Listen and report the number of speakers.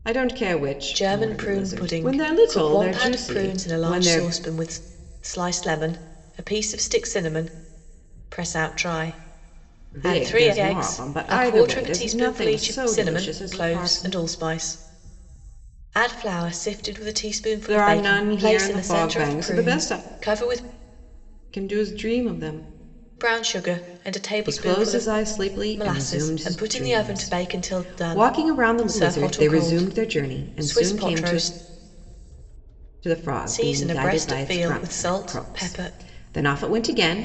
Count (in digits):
2